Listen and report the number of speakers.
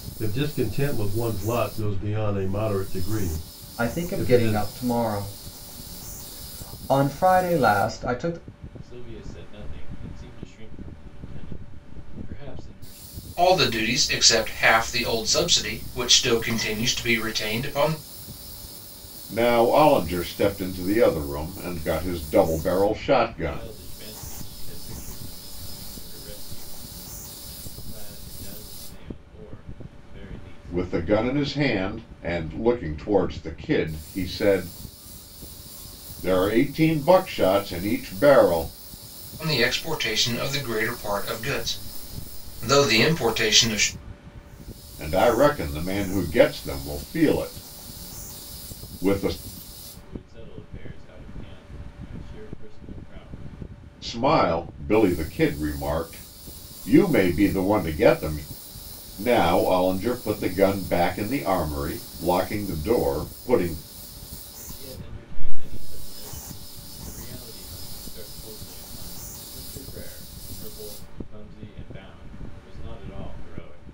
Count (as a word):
five